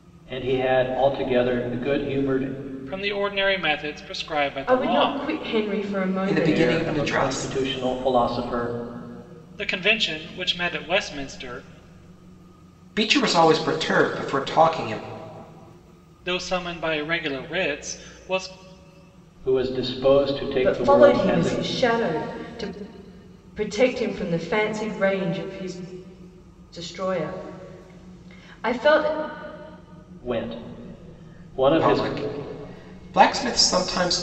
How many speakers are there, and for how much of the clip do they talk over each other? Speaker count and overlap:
4, about 10%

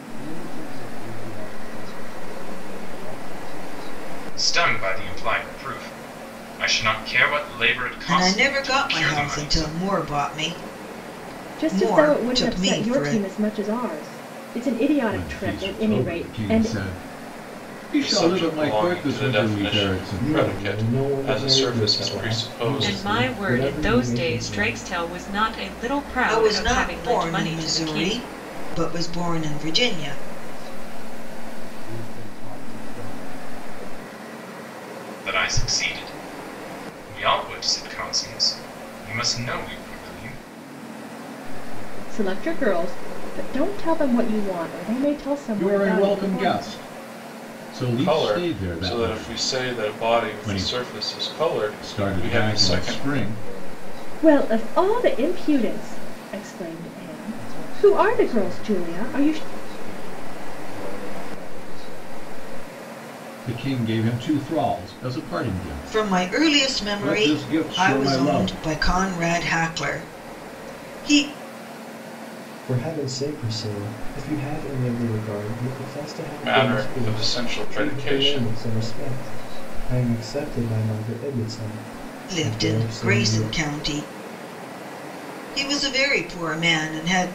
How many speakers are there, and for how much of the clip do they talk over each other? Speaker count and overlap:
8, about 41%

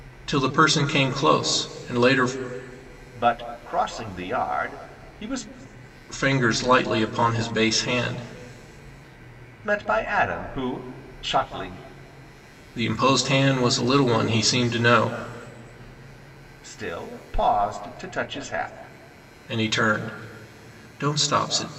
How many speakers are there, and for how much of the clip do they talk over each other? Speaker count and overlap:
2, no overlap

